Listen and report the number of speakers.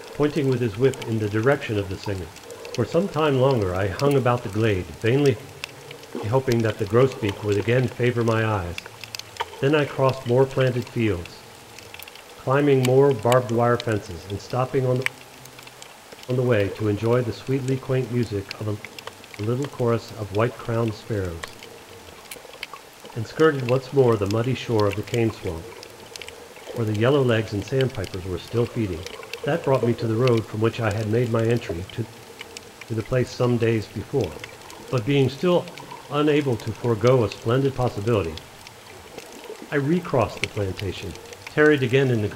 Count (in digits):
1